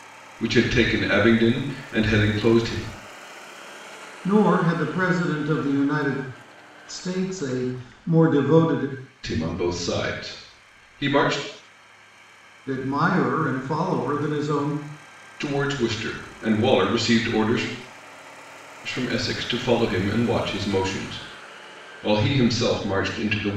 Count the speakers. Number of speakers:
two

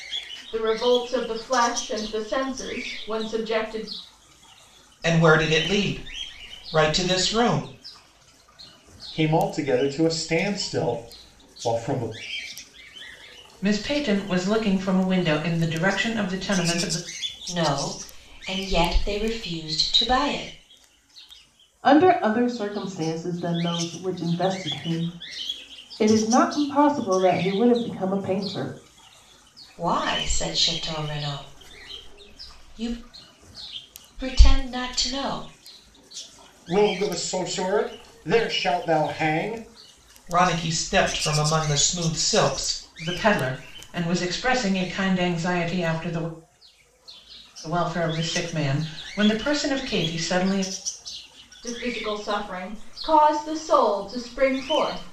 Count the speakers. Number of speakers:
six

